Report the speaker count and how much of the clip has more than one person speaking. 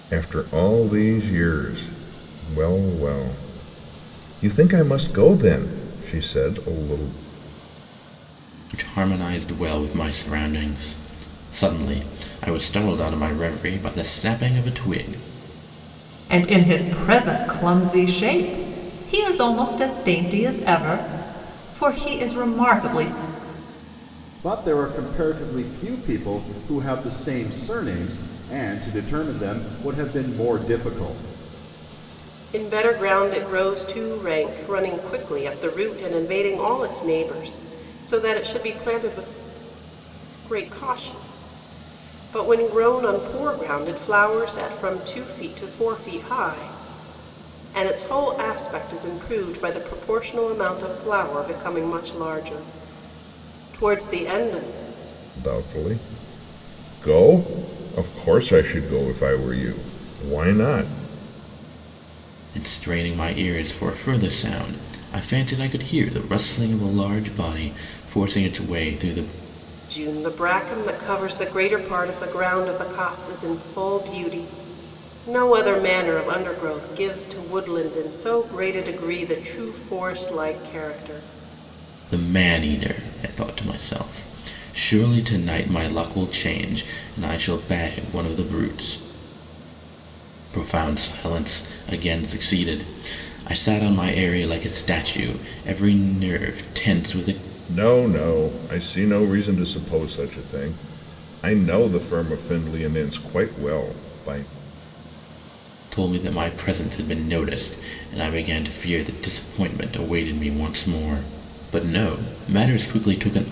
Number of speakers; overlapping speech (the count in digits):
5, no overlap